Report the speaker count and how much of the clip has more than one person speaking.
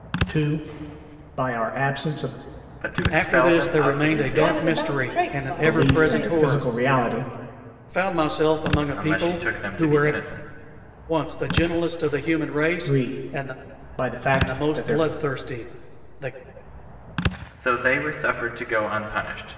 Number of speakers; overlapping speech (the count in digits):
4, about 32%